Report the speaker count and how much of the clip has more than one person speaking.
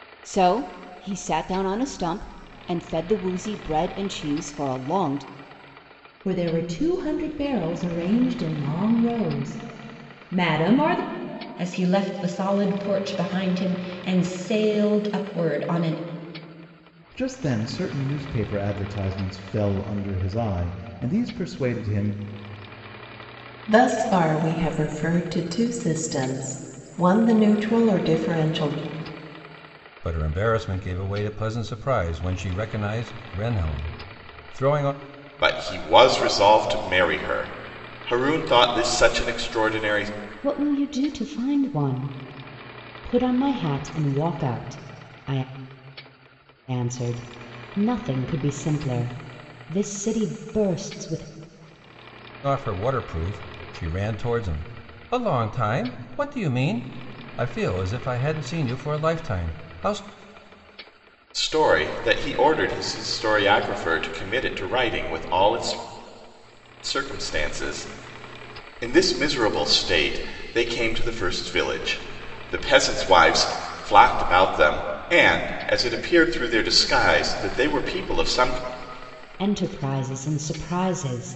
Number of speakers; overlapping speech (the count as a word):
eight, no overlap